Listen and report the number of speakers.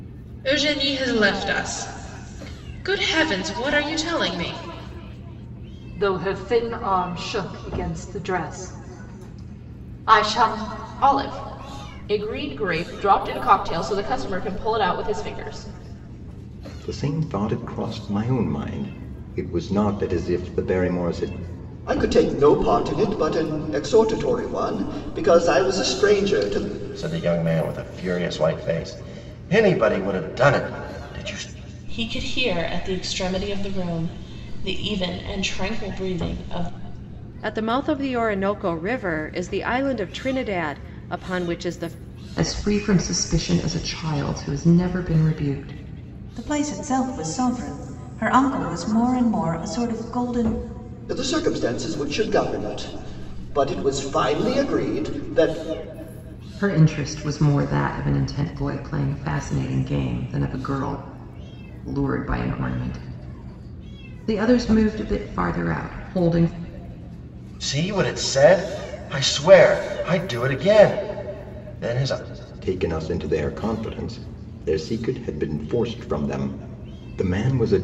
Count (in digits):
10